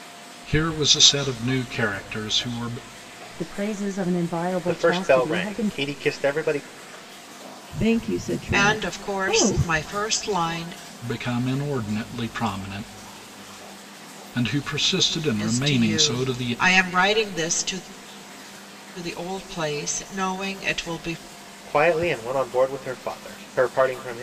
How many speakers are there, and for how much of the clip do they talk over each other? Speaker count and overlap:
5, about 15%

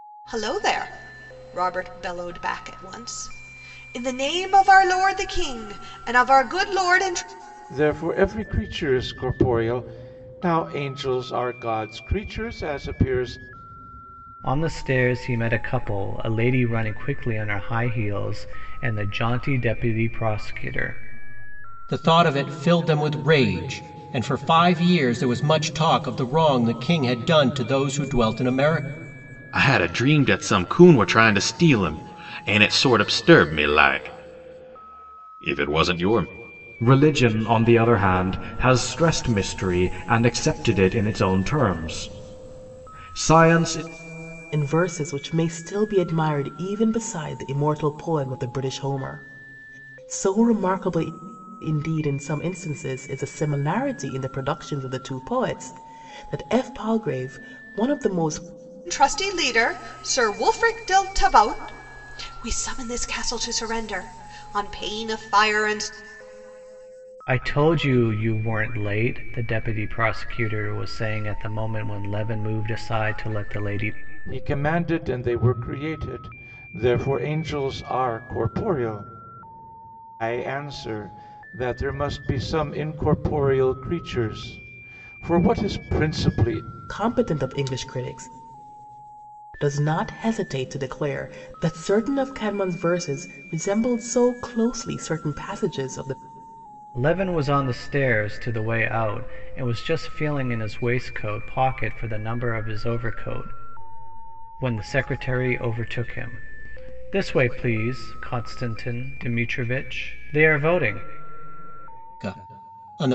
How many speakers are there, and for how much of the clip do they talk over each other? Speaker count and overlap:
7, no overlap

